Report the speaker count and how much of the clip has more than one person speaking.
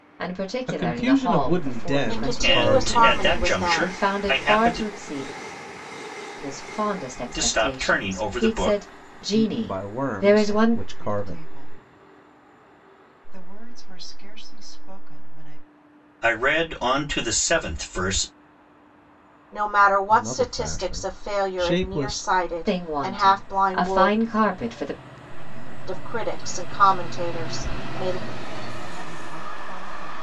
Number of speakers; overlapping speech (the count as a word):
five, about 47%